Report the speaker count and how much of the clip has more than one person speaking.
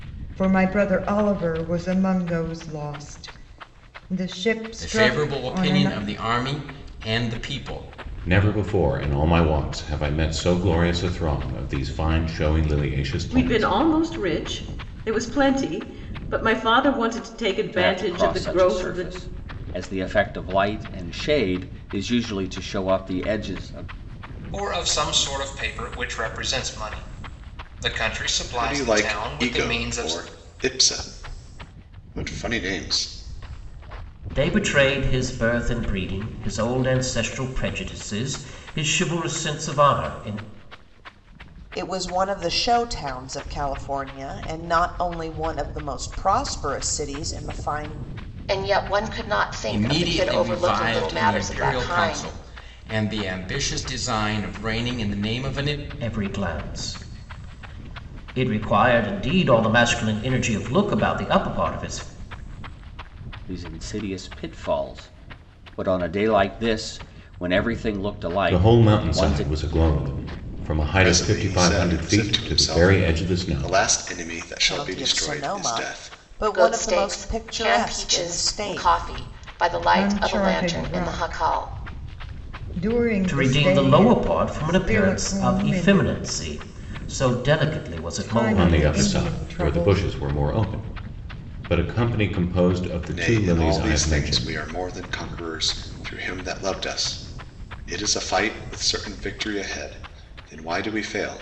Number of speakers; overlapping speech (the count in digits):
10, about 24%